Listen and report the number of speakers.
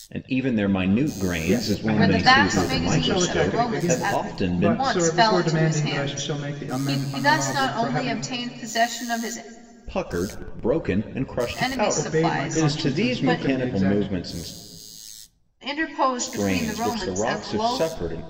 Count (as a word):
three